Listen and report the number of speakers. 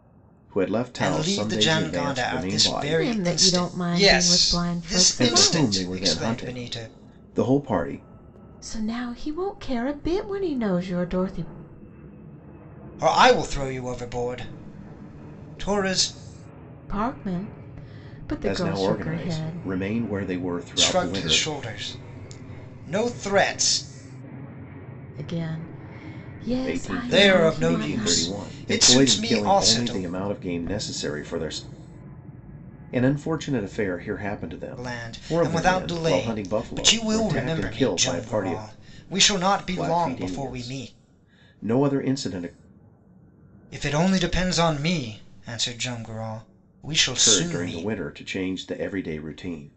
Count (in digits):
3